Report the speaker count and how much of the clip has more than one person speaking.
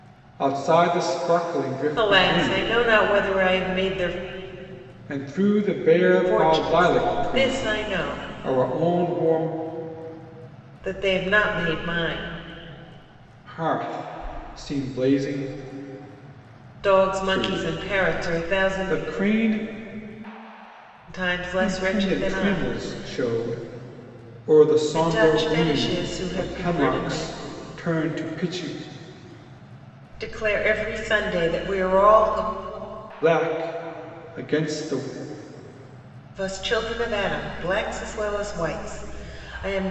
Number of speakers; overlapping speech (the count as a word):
two, about 21%